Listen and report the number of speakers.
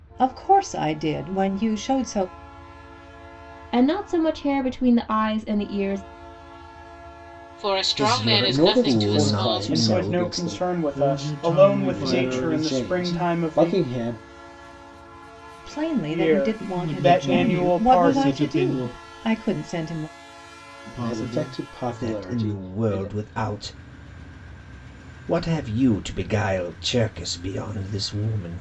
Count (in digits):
7